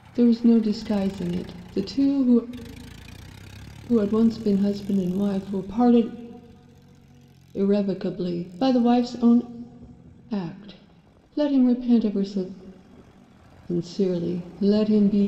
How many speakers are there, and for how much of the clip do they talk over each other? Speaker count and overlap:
one, no overlap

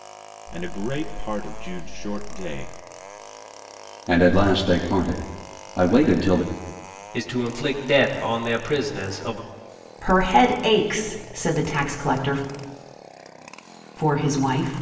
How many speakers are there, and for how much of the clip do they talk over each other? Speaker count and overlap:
four, no overlap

